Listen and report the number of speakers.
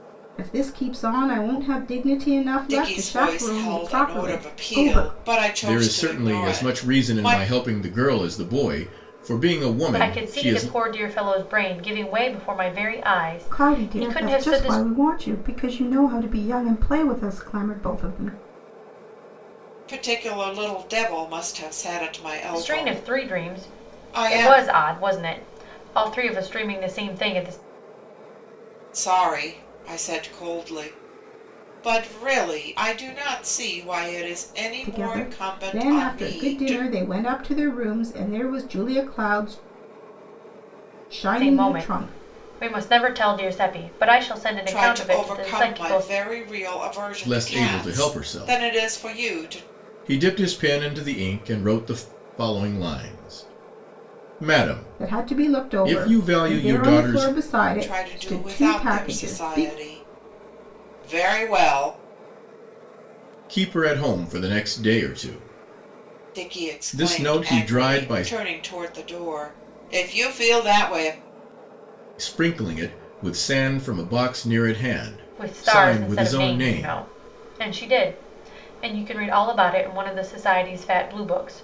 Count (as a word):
four